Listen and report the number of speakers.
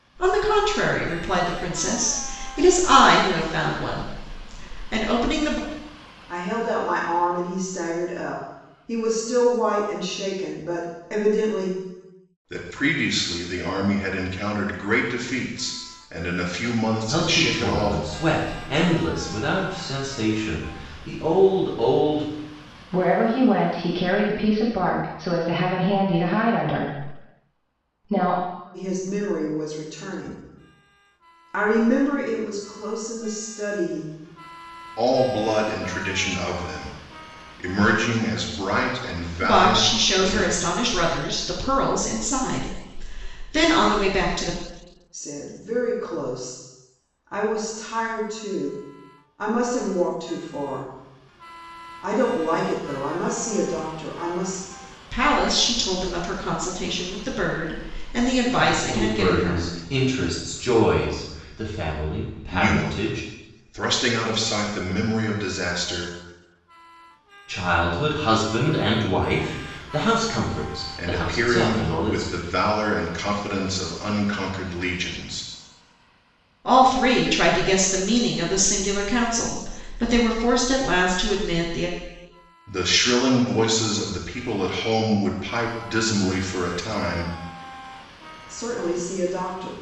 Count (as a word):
five